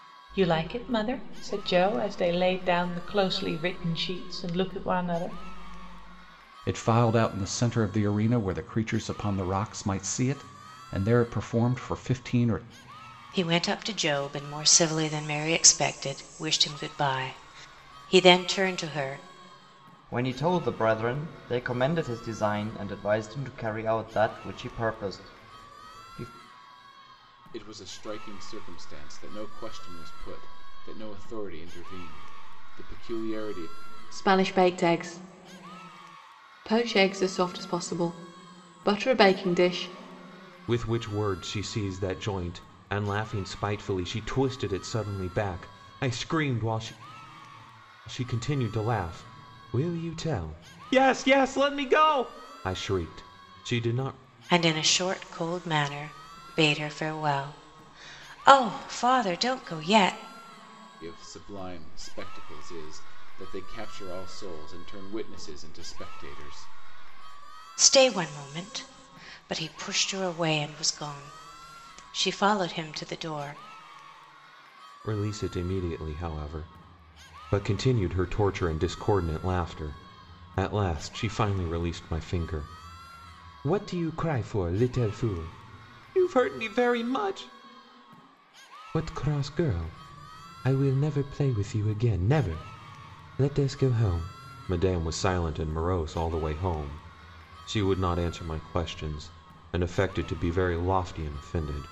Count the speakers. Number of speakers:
7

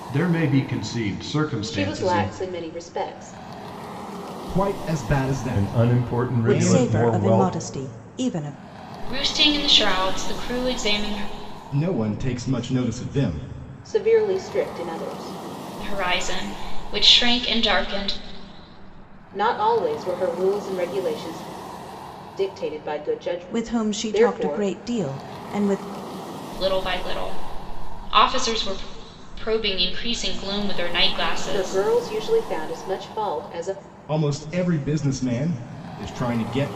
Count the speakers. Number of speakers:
6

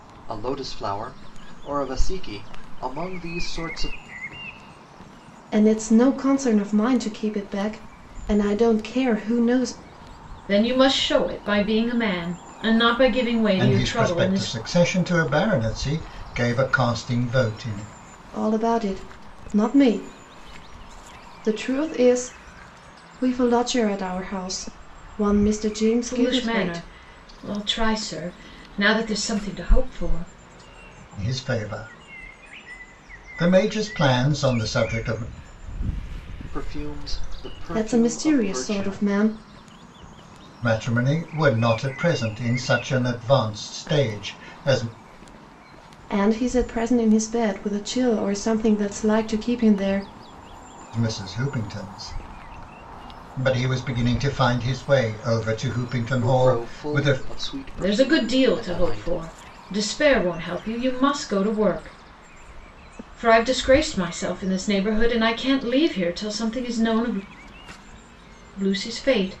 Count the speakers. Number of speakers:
4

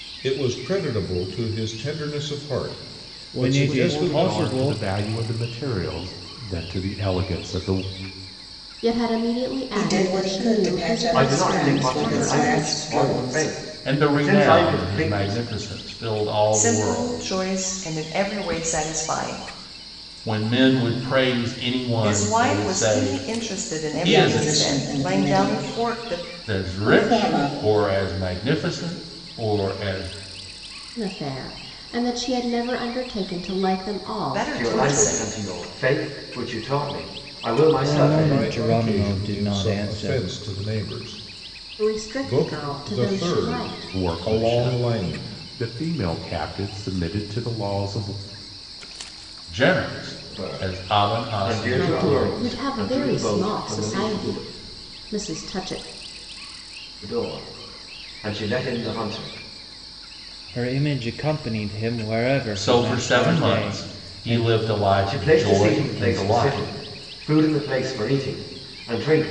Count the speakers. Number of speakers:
8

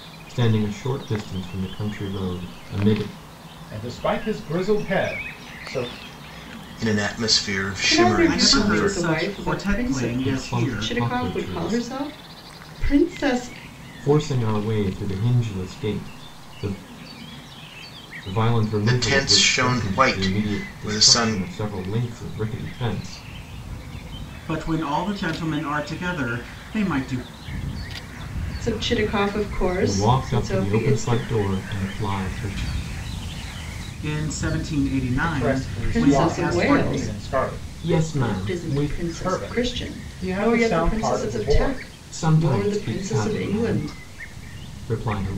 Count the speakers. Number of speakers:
5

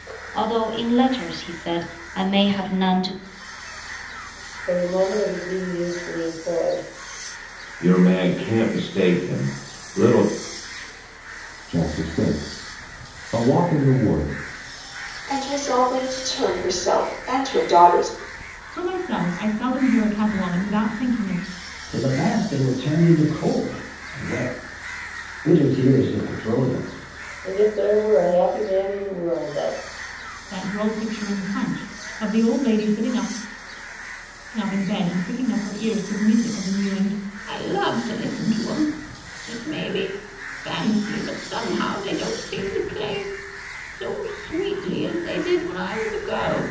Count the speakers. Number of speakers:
7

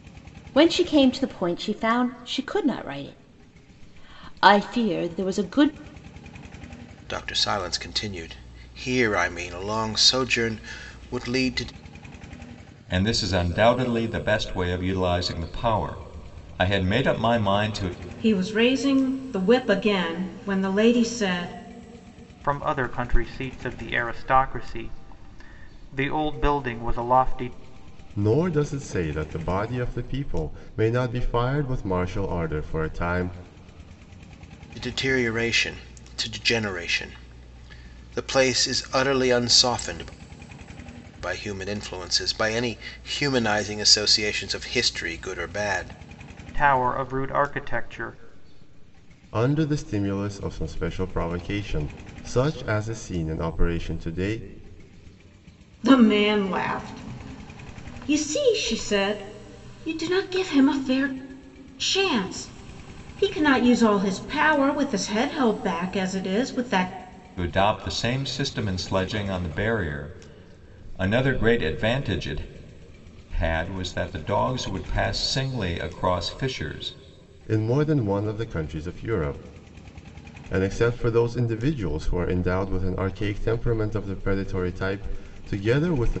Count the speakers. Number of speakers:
6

